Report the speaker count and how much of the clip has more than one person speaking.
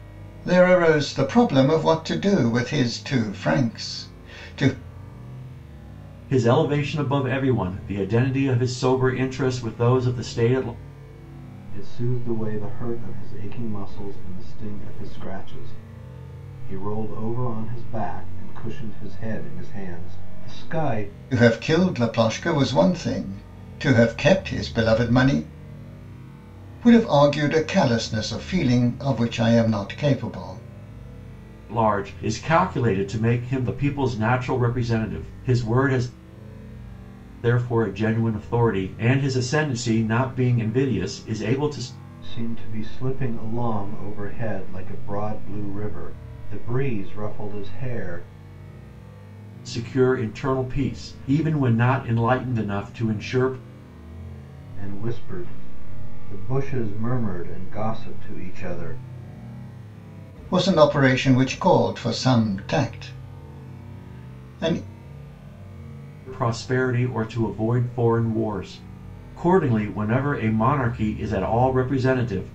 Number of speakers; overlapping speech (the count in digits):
3, no overlap